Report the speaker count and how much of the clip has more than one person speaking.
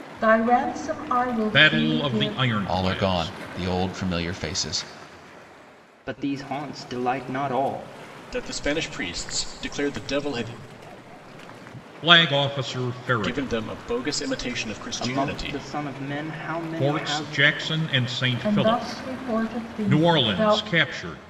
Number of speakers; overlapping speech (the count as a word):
five, about 23%